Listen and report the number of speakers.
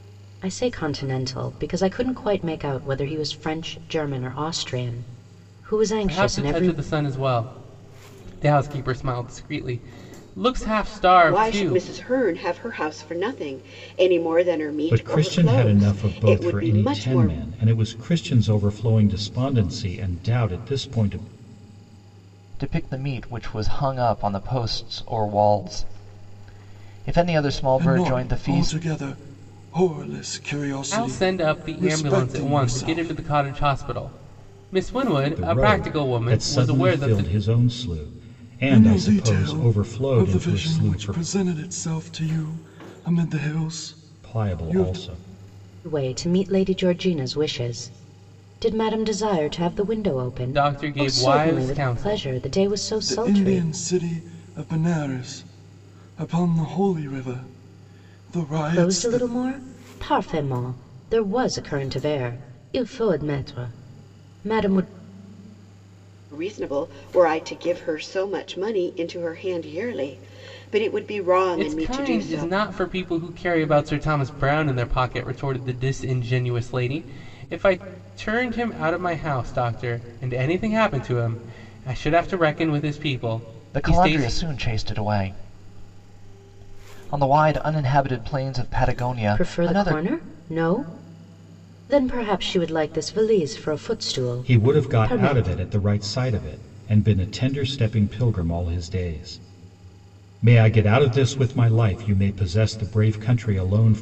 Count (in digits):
6